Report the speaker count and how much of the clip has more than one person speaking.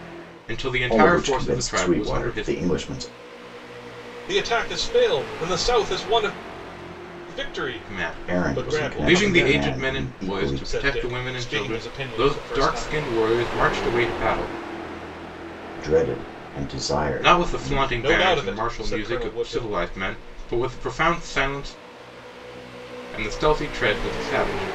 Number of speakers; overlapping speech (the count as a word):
three, about 39%